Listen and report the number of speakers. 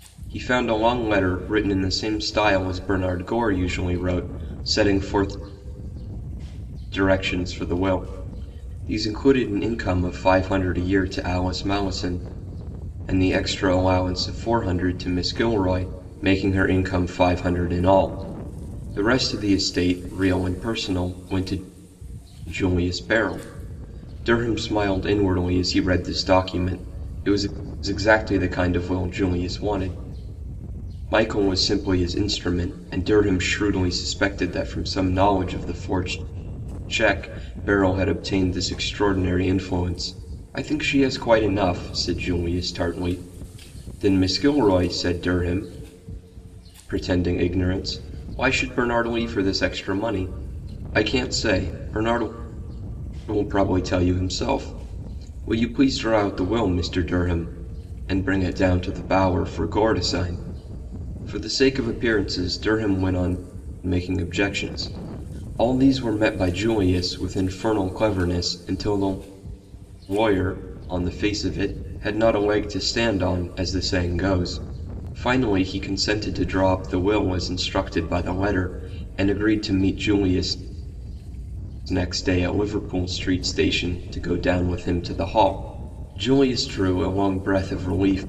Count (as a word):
one